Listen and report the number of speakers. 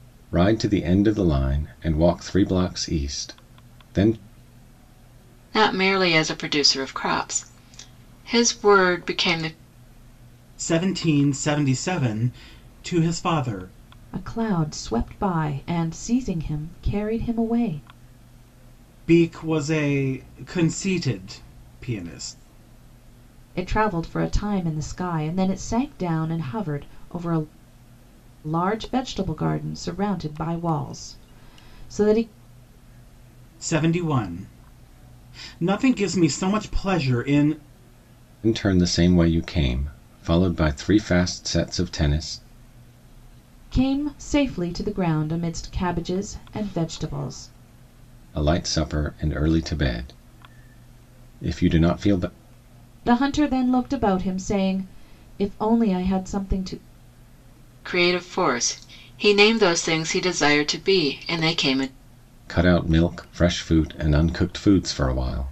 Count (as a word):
four